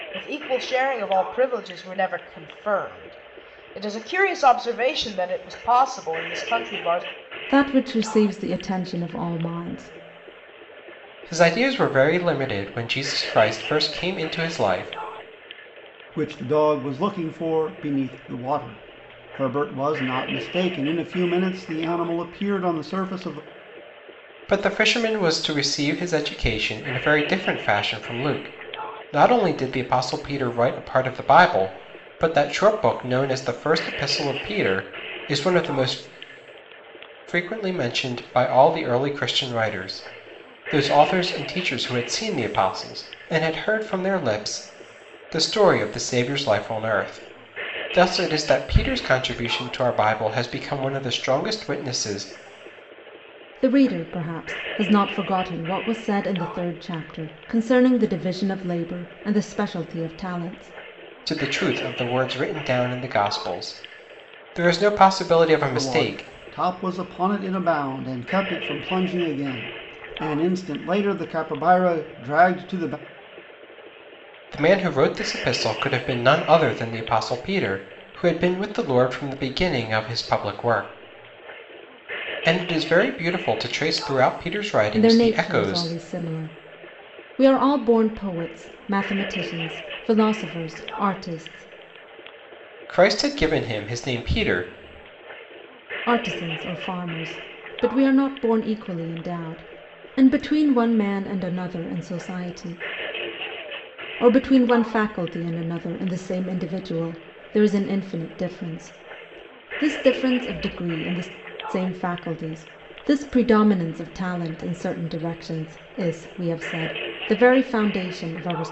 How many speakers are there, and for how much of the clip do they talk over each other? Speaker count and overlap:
4, about 1%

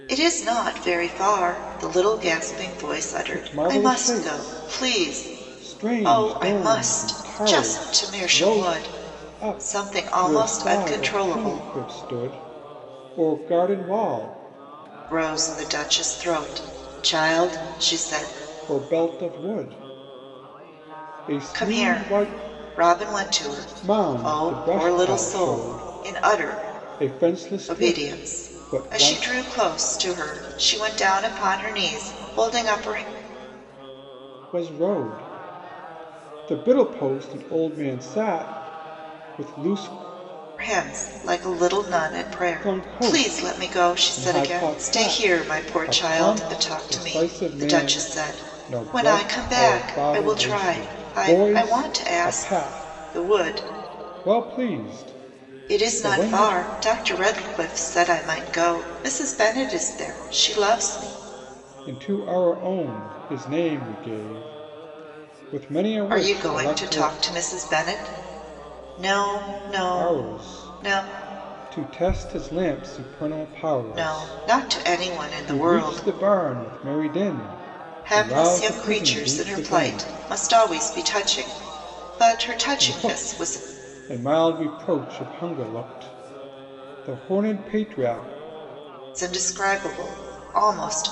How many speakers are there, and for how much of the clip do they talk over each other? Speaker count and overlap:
2, about 34%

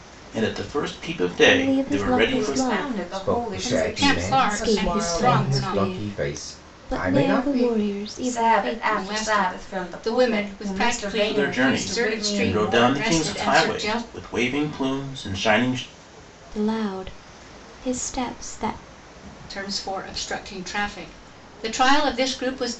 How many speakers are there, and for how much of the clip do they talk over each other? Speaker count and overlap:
5, about 50%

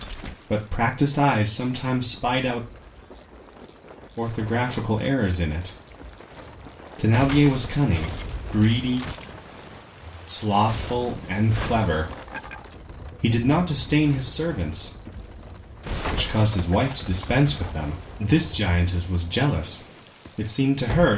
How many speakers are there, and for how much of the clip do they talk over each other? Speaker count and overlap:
1, no overlap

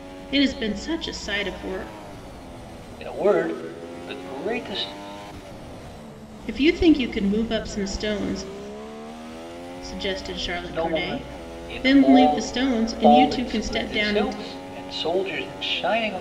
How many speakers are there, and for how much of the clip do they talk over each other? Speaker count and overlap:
2, about 20%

